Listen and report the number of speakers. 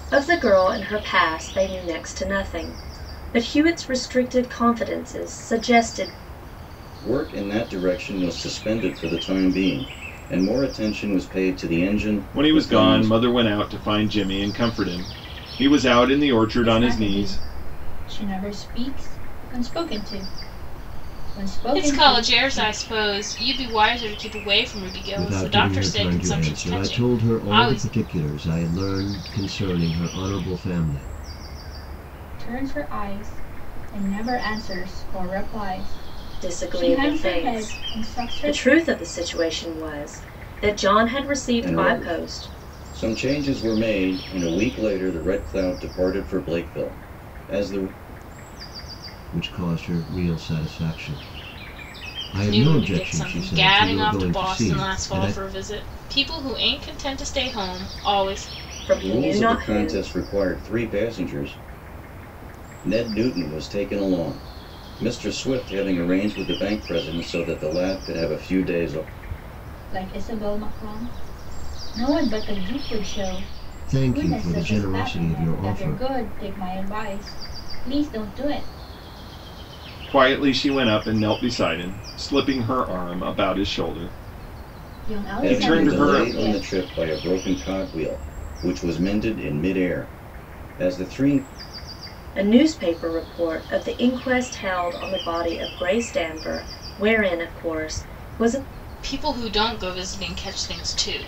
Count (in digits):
6